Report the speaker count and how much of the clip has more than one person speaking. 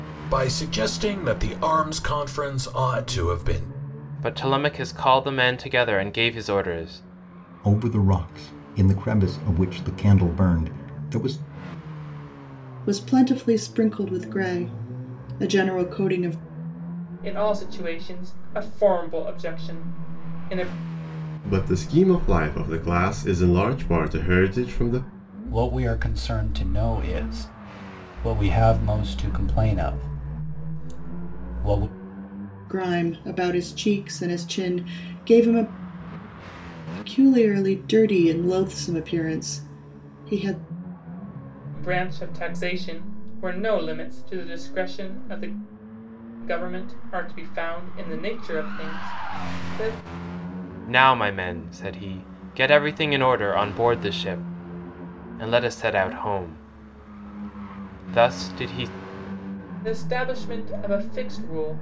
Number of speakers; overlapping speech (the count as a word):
seven, no overlap